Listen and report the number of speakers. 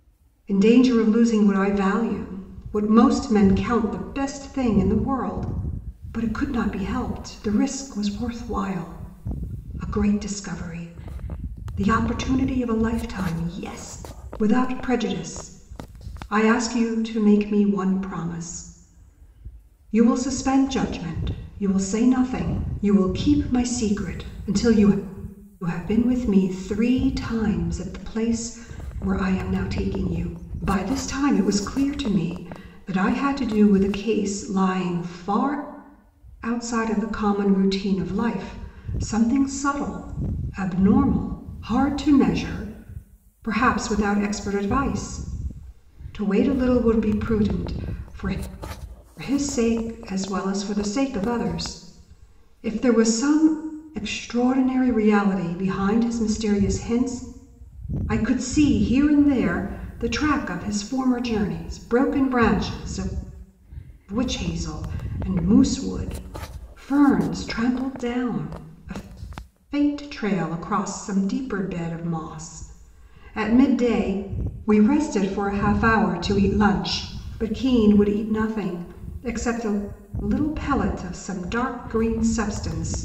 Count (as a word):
one